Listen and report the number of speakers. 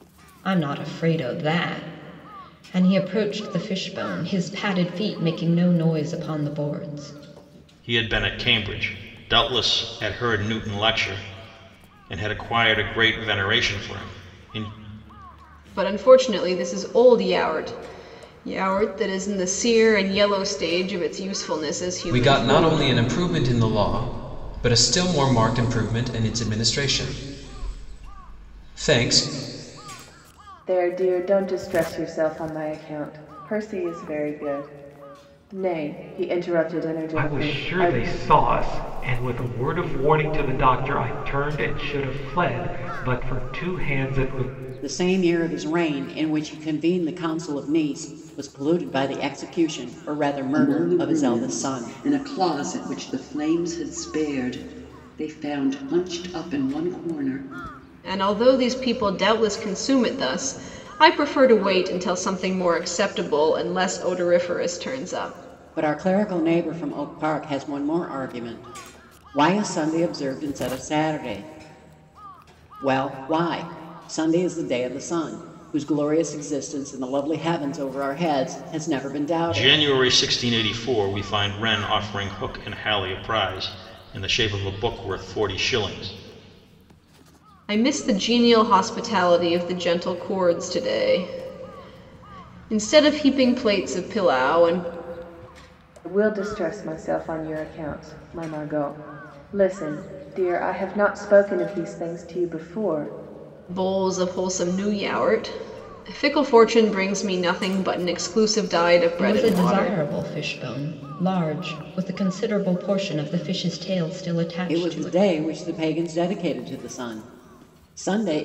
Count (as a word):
eight